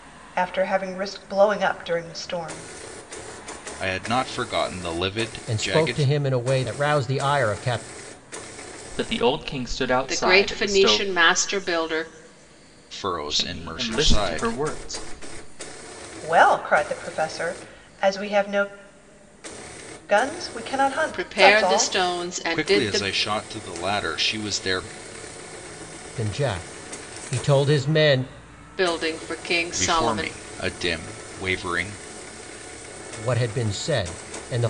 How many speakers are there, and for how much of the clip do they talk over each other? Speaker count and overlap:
5, about 15%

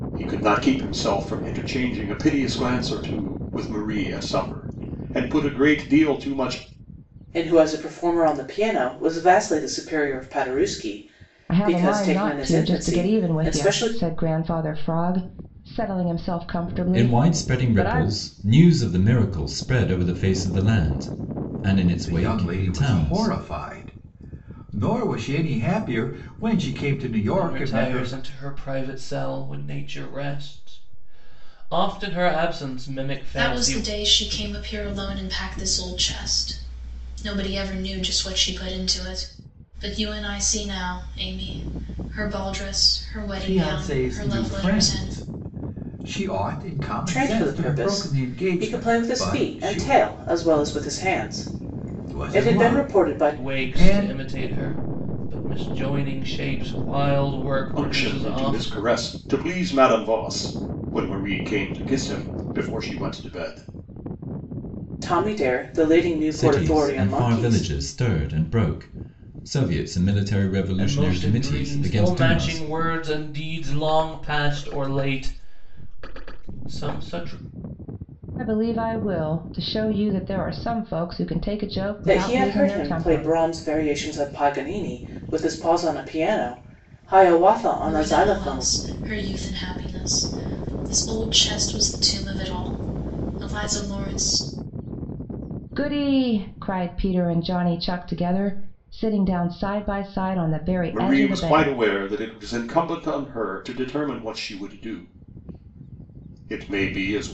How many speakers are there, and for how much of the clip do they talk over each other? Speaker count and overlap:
7, about 19%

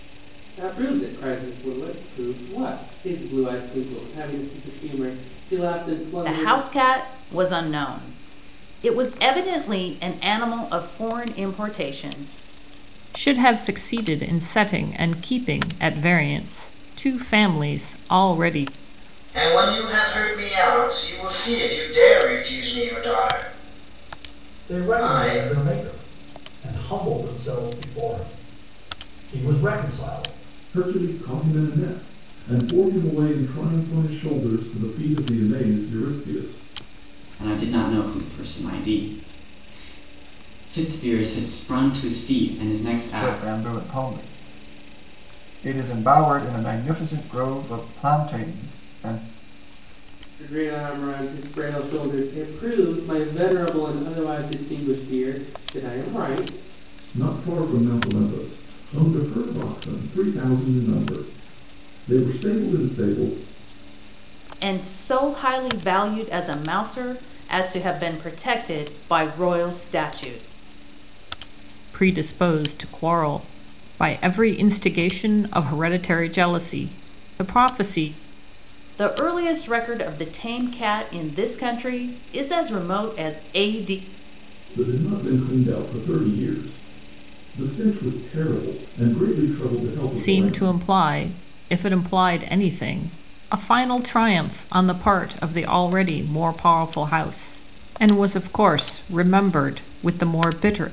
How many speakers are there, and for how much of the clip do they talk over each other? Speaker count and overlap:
8, about 2%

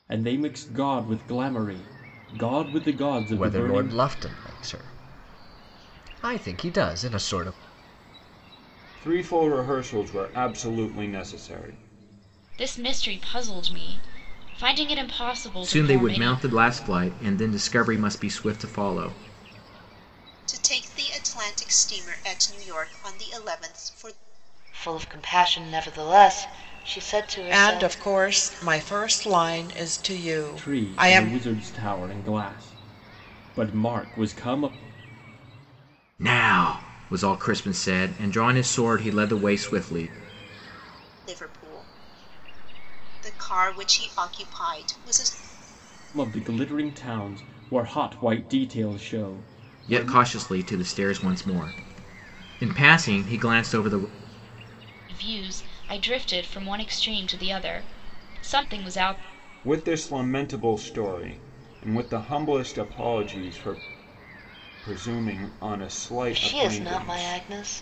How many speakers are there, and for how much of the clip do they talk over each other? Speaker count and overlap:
8, about 6%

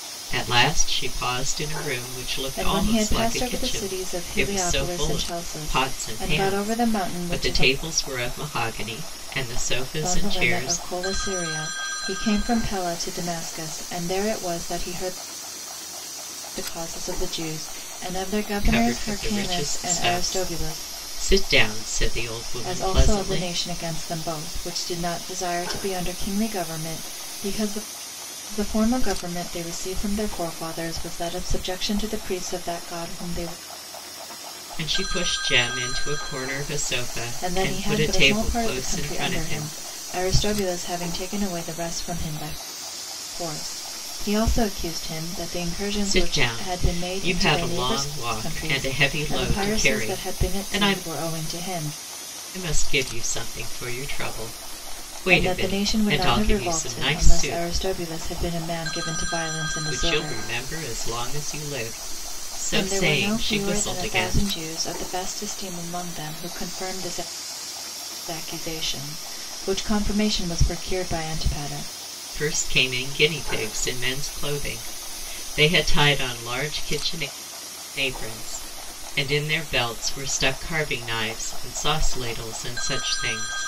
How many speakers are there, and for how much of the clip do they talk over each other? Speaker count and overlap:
2, about 25%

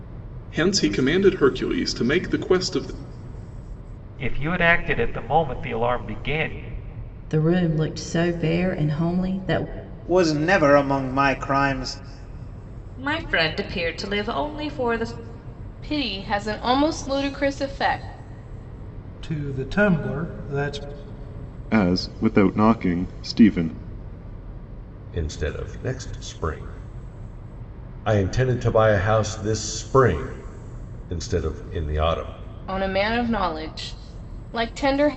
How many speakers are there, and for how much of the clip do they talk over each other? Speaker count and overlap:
9, no overlap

